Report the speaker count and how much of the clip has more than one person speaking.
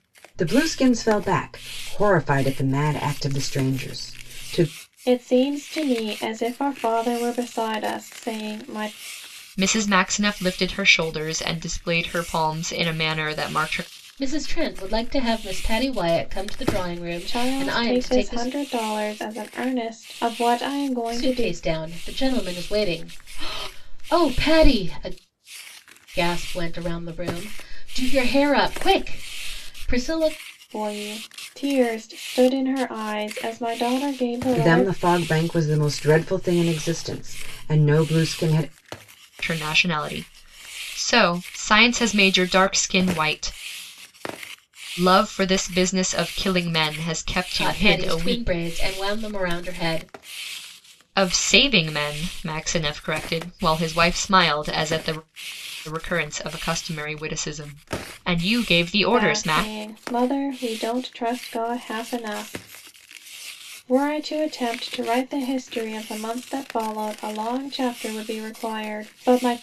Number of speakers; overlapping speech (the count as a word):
four, about 6%